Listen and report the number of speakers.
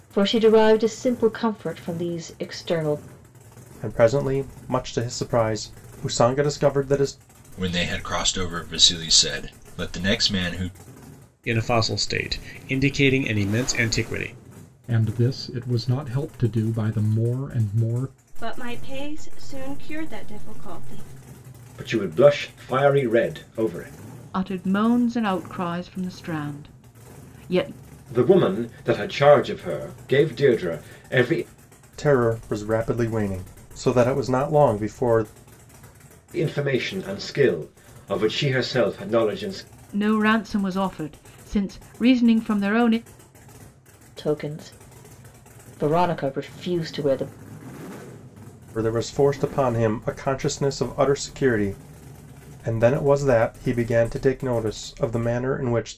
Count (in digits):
8